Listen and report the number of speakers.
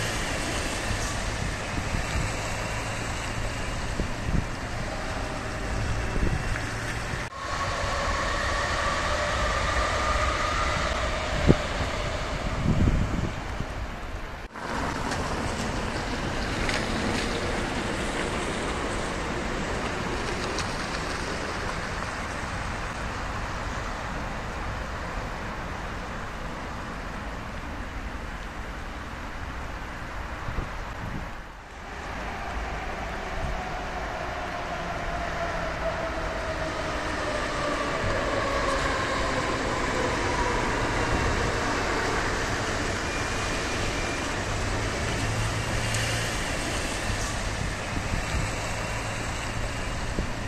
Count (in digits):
0